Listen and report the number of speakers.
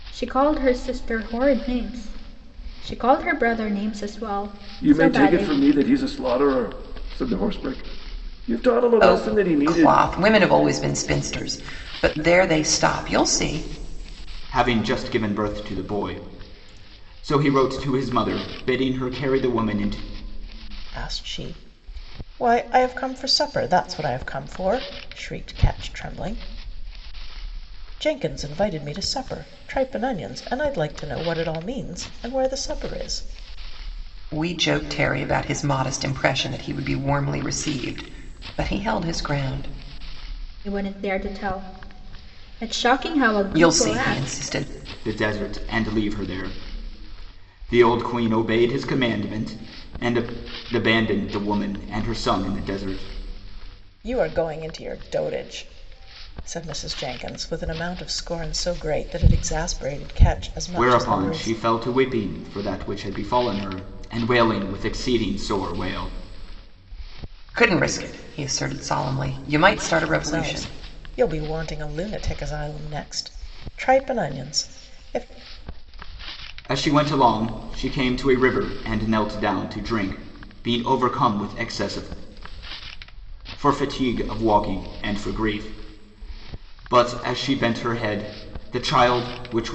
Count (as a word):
five